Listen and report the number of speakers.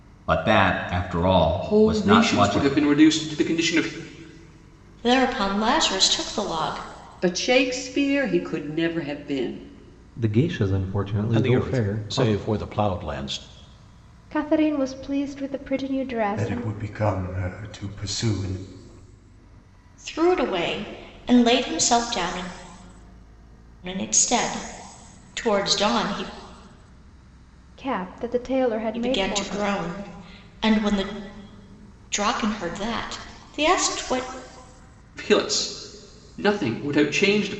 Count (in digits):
8